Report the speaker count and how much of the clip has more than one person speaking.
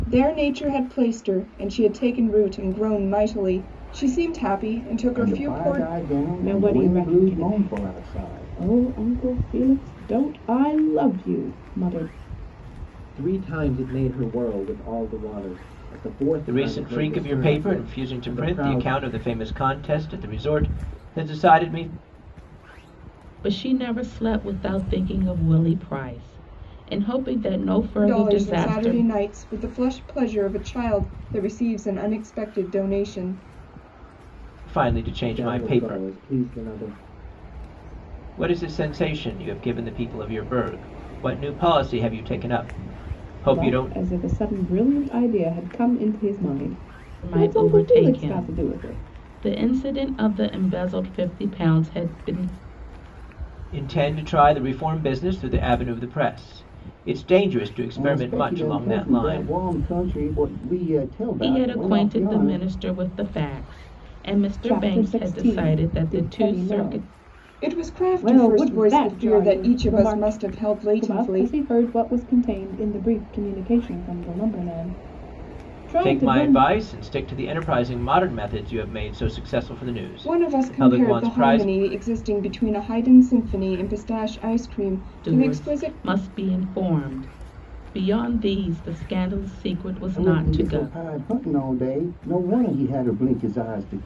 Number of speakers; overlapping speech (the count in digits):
6, about 24%